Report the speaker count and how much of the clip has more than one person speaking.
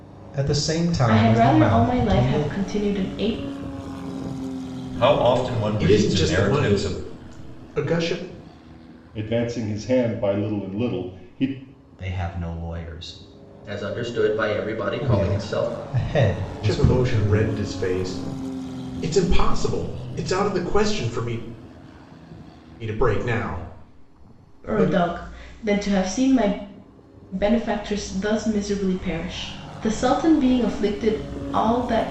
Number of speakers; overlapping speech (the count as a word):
seven, about 14%